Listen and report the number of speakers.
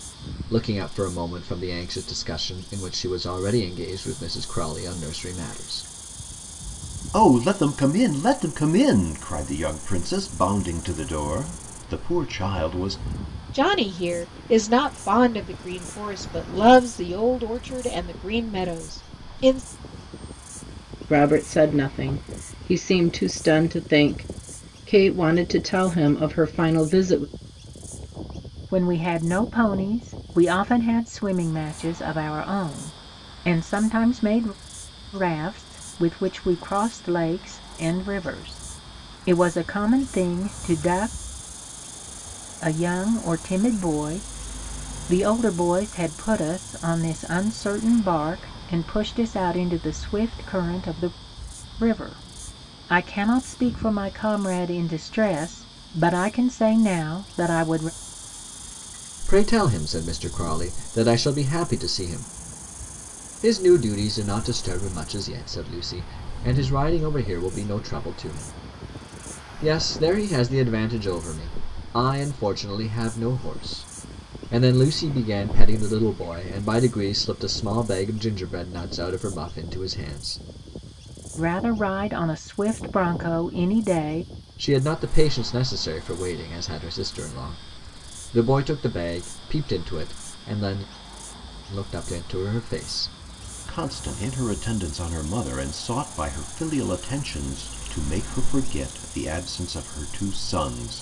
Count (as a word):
five